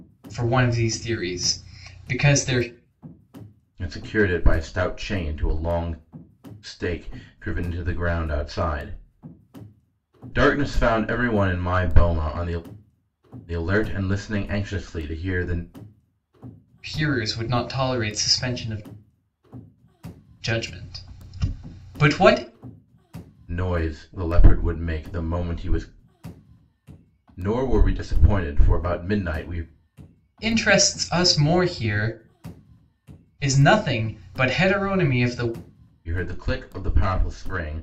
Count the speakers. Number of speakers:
2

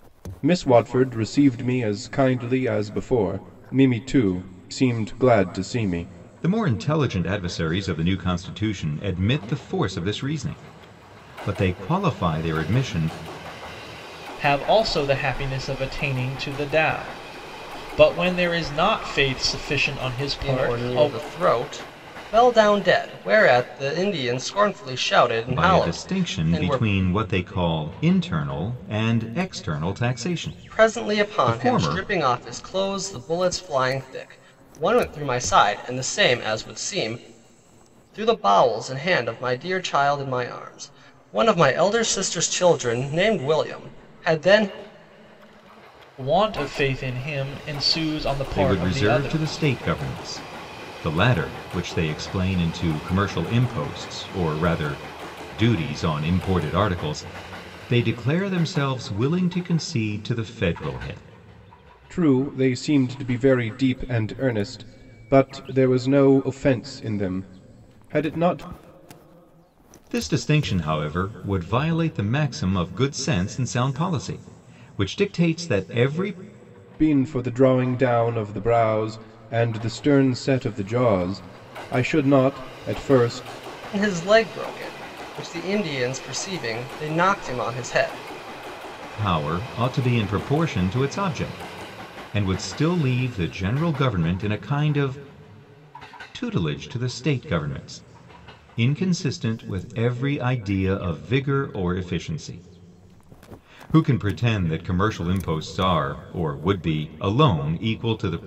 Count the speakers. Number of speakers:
4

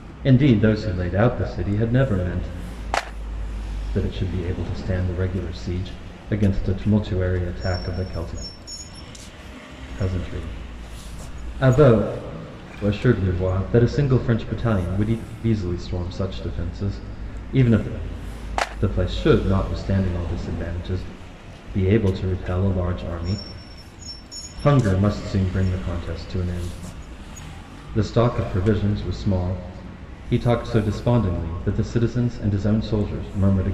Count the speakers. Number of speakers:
1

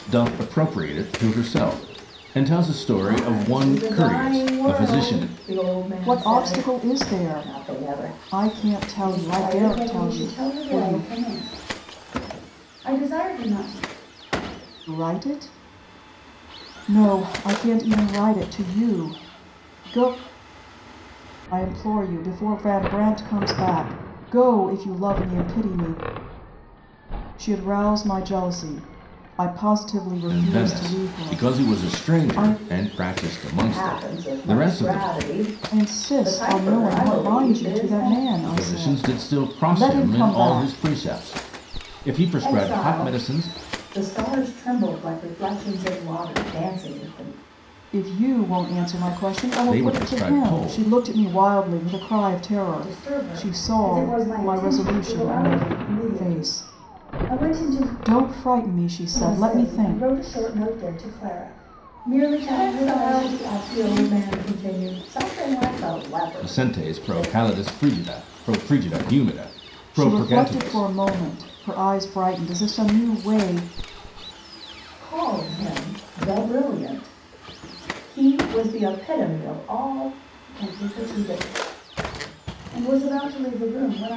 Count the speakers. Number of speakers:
4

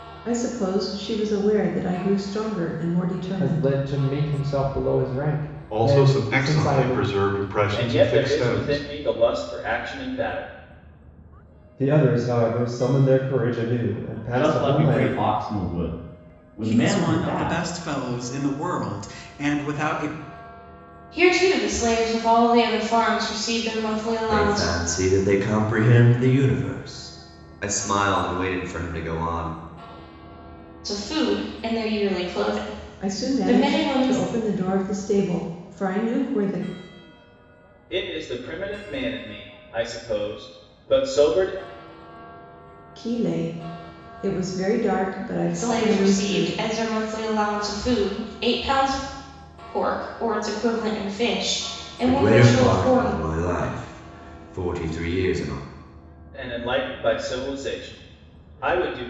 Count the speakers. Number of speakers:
9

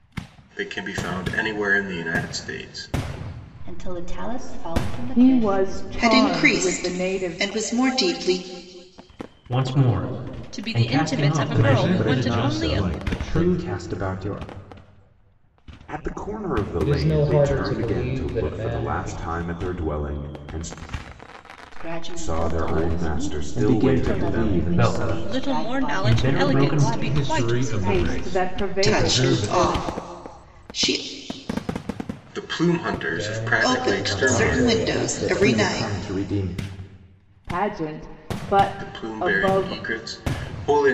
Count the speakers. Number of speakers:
10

